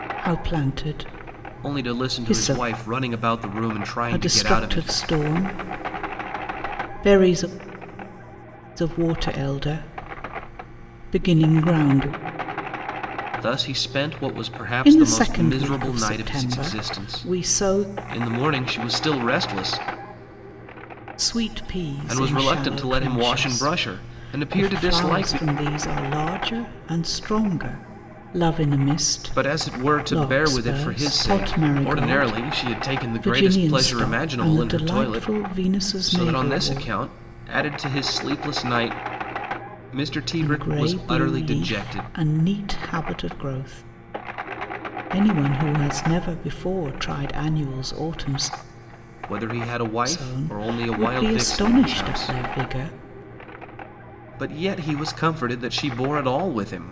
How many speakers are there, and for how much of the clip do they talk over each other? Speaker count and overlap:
2, about 34%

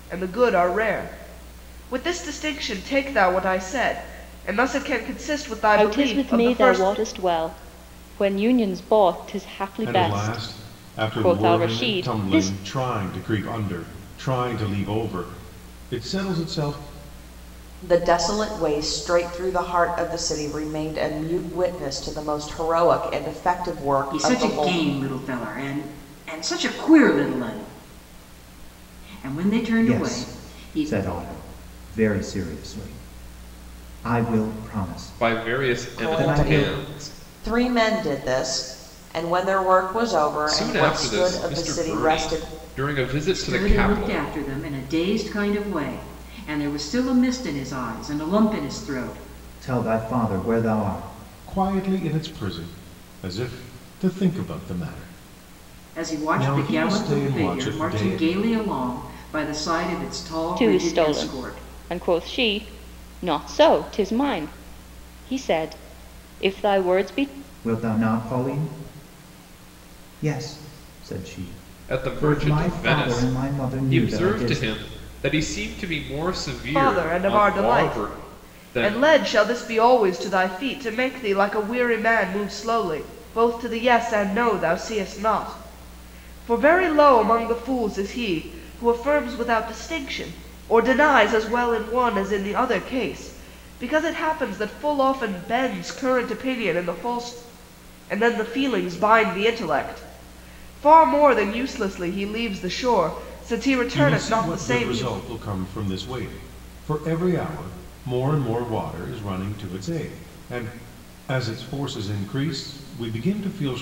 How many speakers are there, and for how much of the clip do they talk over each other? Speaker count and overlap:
7, about 18%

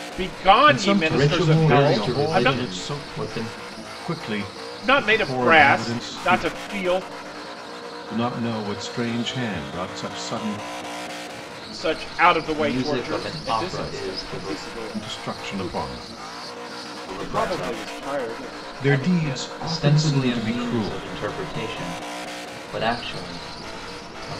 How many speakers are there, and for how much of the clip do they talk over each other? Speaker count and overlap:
3, about 40%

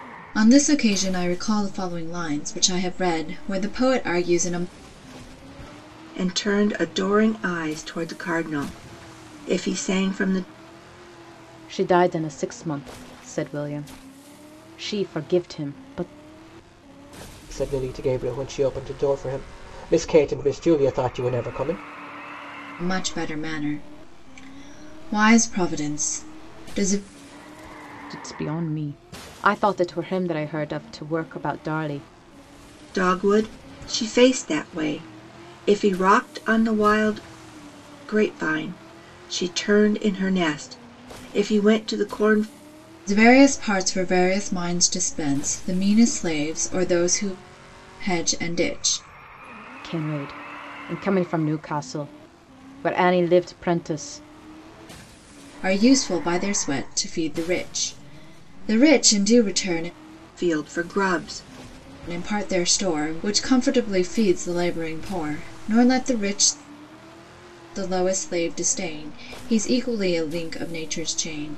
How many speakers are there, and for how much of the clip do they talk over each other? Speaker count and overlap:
4, no overlap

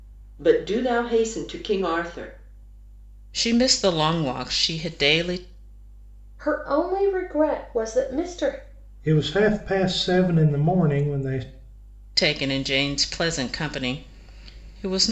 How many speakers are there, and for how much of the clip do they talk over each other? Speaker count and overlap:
4, no overlap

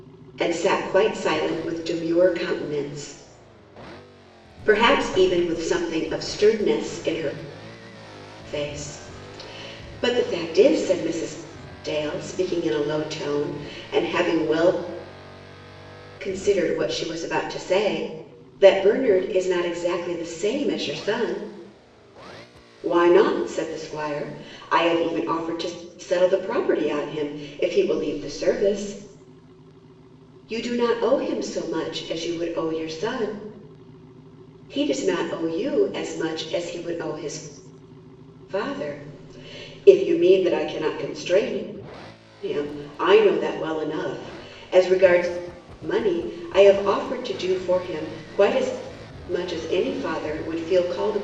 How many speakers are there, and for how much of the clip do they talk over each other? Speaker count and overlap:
1, no overlap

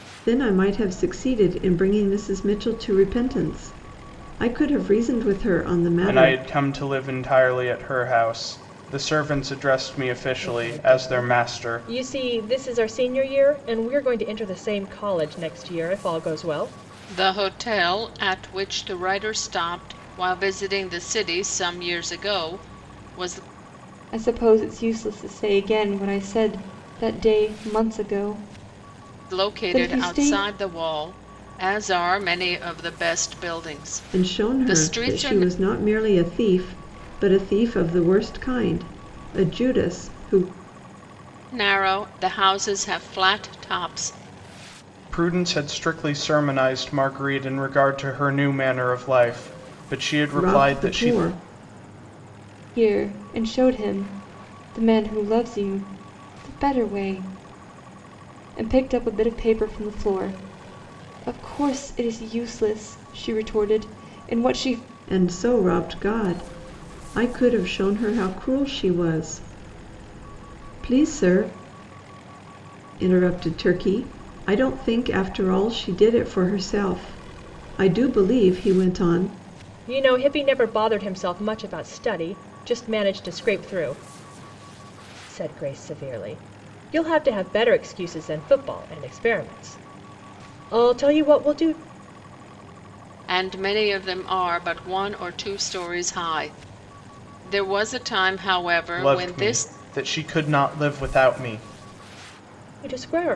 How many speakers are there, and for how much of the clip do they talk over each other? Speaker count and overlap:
5, about 6%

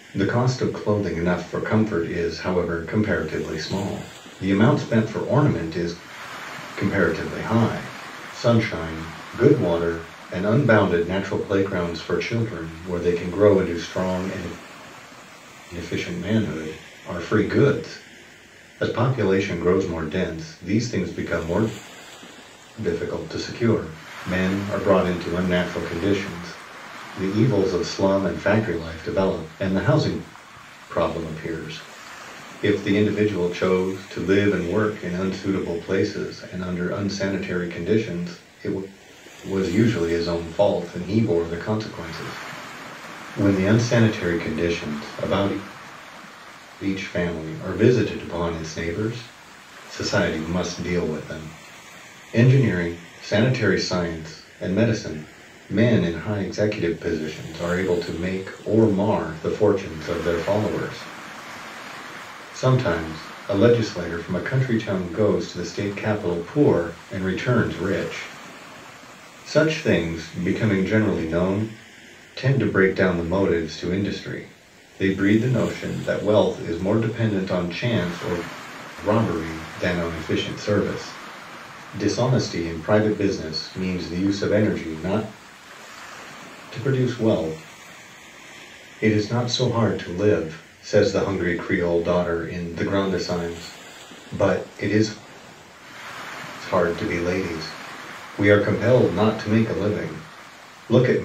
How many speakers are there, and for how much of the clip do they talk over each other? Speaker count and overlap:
1, no overlap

